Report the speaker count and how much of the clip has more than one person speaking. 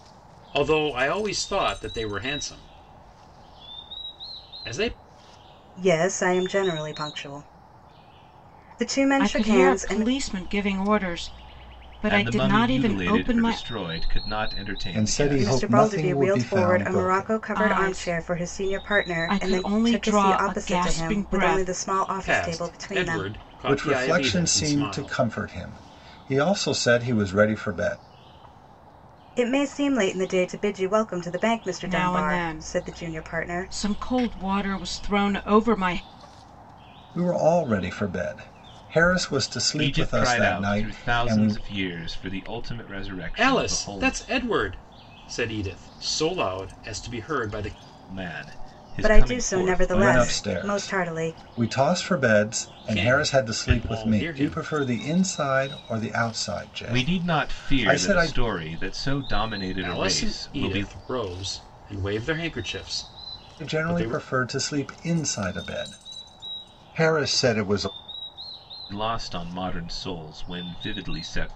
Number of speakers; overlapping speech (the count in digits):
5, about 33%